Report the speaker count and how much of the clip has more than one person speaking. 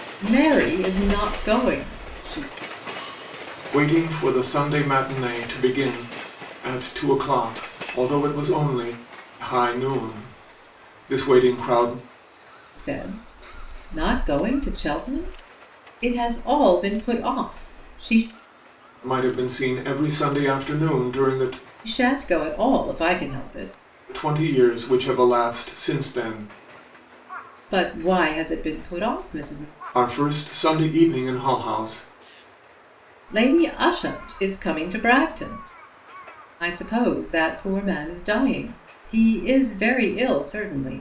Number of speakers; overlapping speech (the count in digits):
2, no overlap